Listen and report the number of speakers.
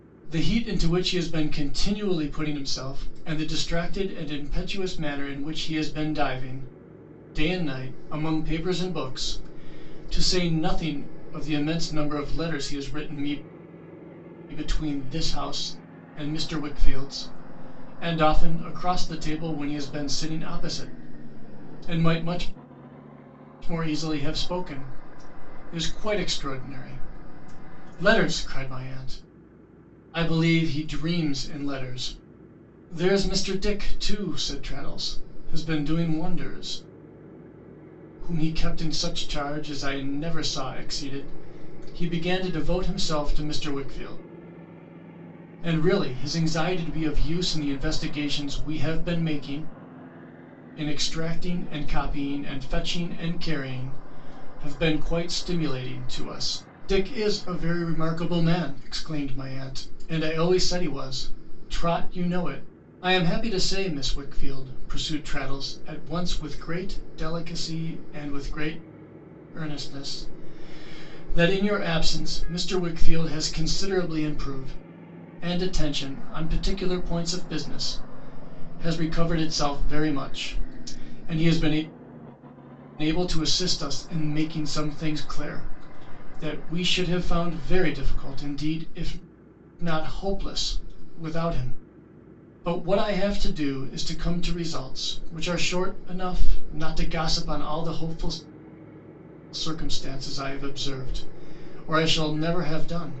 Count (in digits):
1